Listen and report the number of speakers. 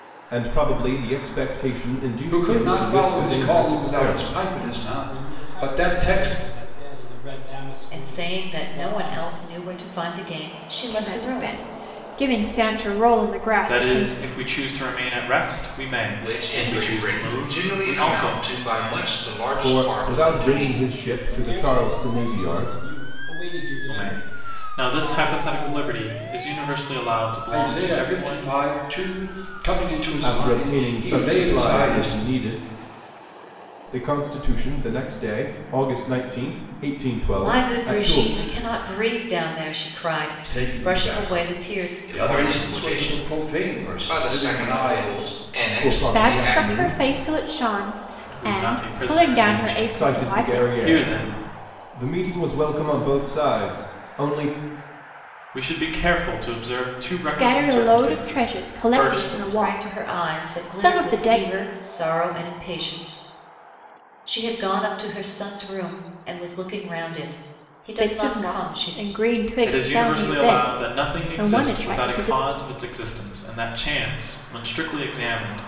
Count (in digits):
7